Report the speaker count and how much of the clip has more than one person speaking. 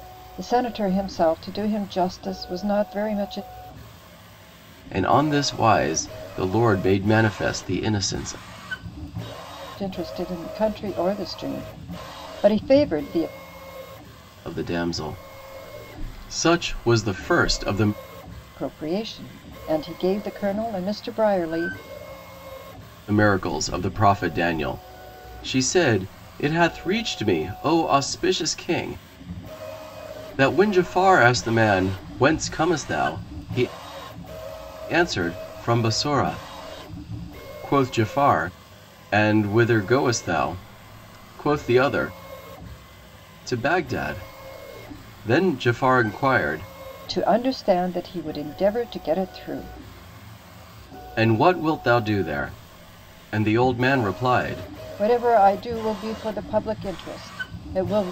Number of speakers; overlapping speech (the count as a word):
two, no overlap